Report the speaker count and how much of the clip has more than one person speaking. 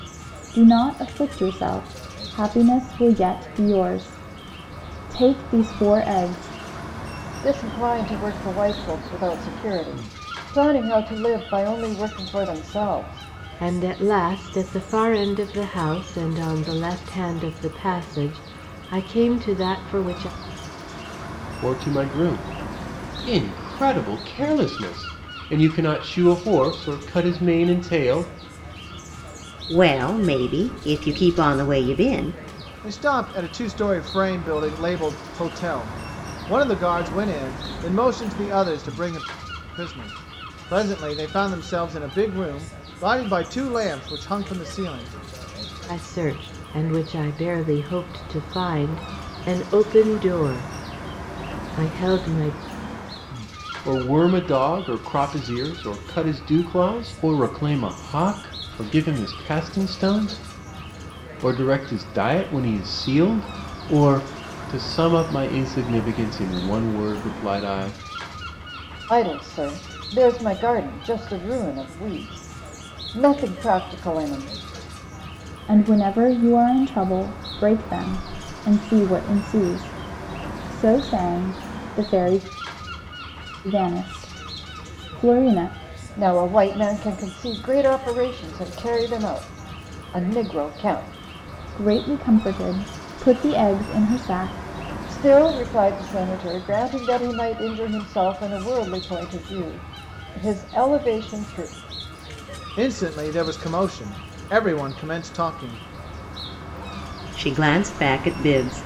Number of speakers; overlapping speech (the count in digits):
6, no overlap